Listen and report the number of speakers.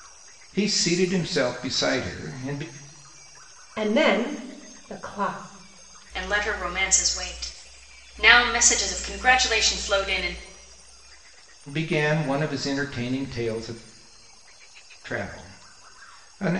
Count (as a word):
three